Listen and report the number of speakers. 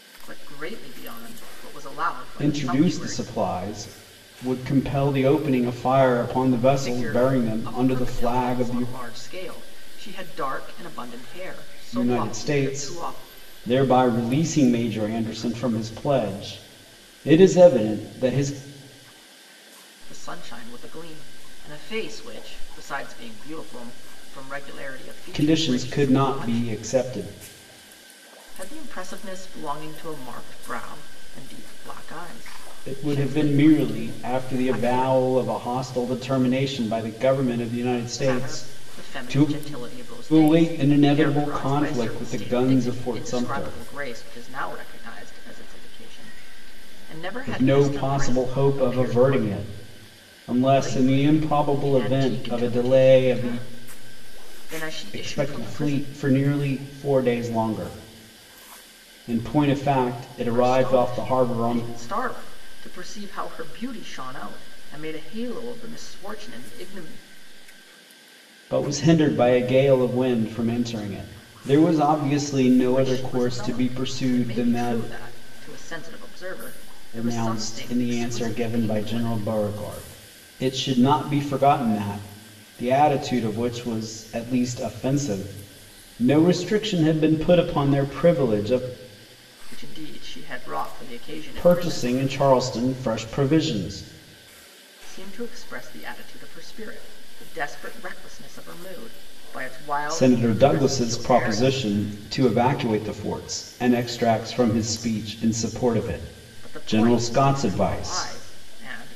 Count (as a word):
two